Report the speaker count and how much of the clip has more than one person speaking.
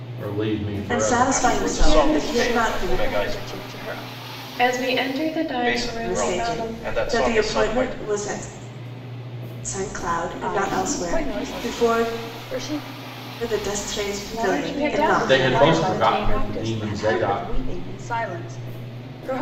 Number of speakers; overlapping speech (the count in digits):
5, about 51%